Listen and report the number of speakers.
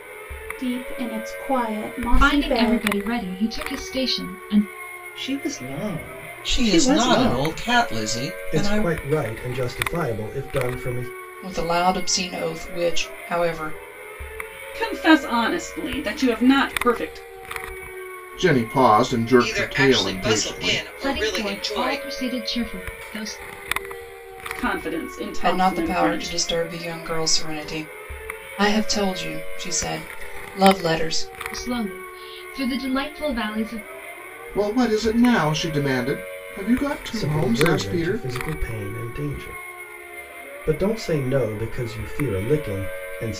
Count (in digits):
9